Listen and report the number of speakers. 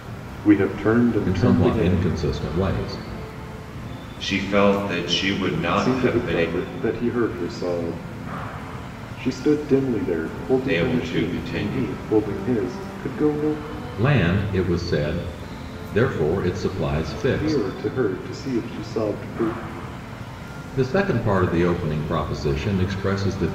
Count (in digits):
3